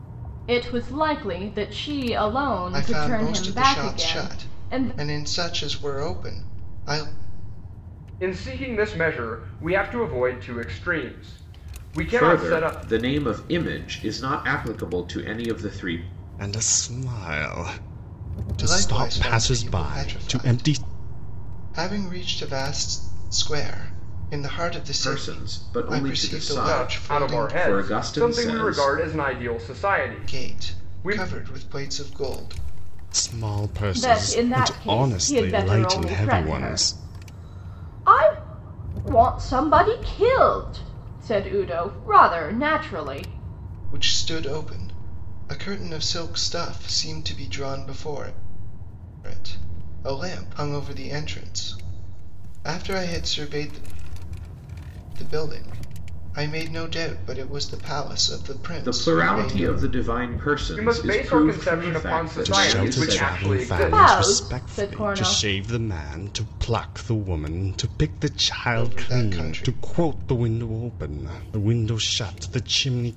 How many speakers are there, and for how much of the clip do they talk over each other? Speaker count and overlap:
five, about 27%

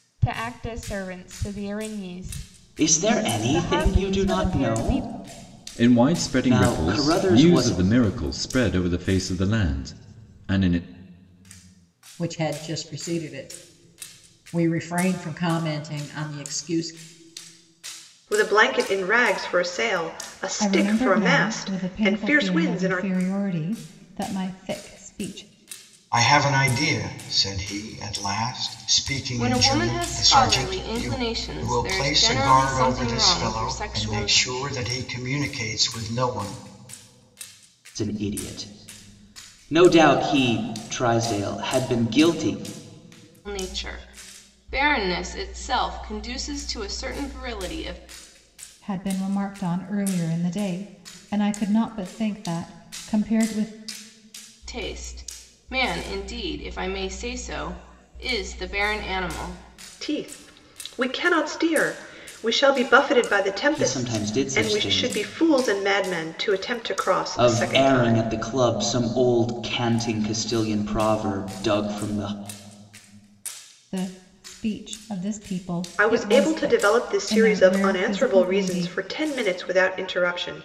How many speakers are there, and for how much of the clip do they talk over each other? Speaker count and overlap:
eight, about 21%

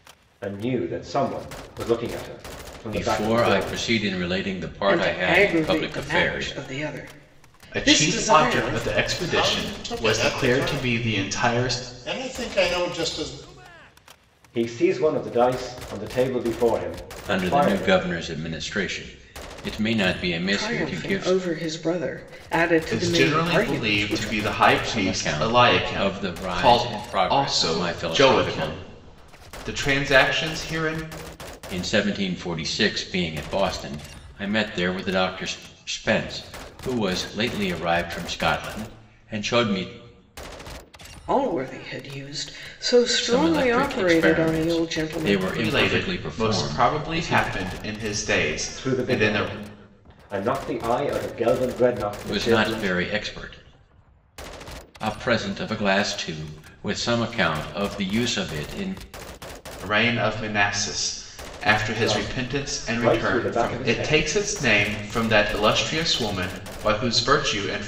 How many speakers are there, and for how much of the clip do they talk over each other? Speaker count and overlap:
five, about 32%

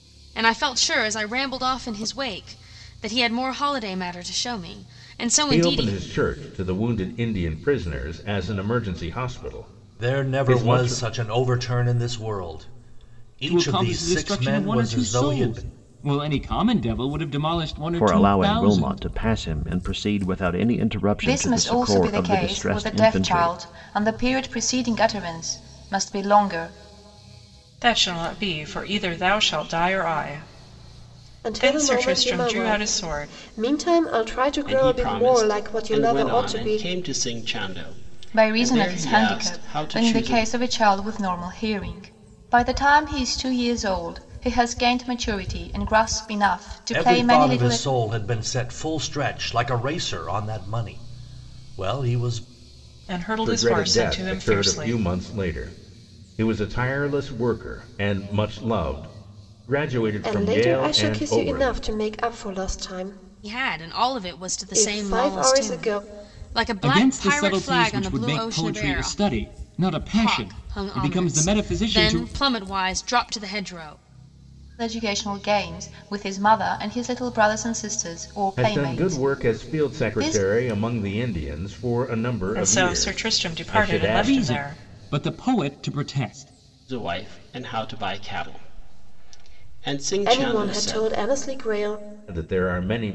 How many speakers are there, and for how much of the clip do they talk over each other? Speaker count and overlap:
nine, about 32%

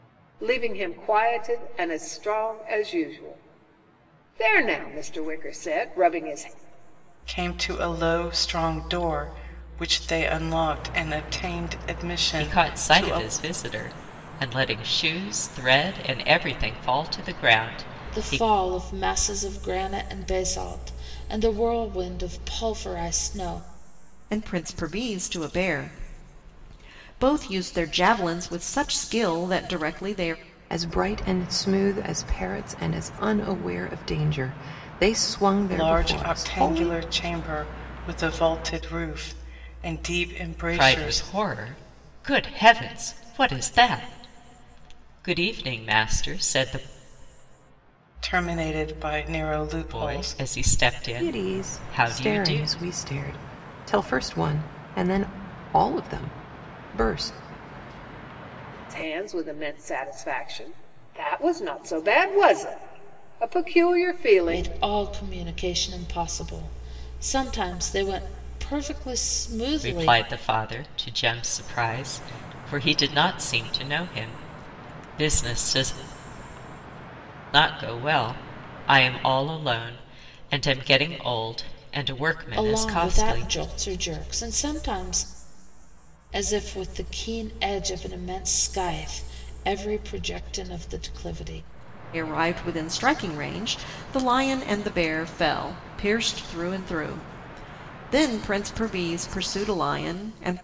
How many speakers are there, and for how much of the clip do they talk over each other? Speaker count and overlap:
six, about 7%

